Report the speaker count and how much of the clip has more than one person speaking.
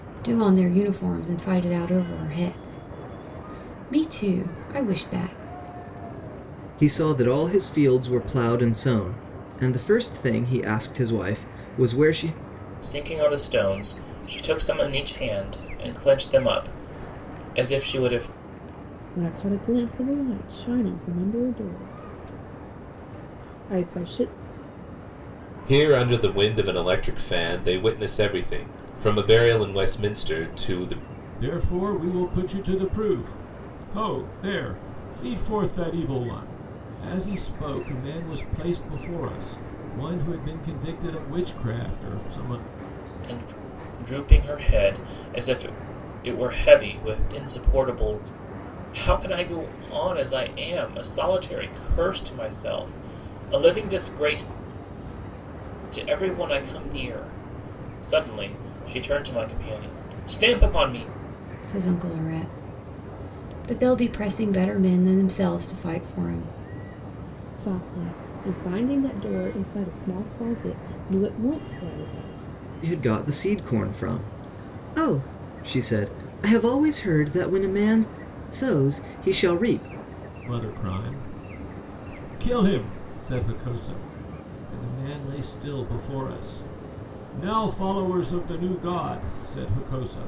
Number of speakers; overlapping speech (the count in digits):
6, no overlap